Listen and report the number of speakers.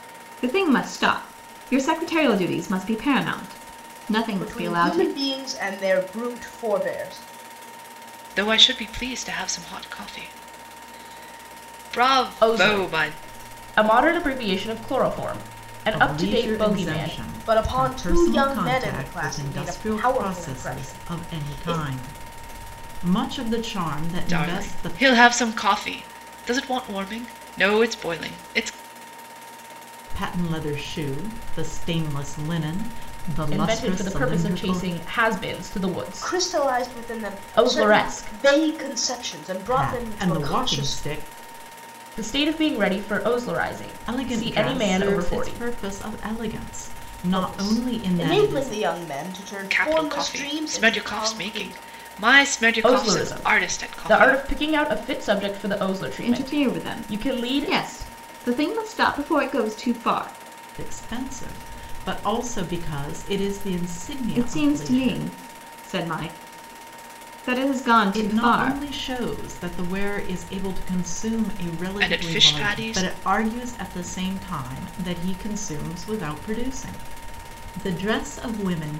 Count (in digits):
5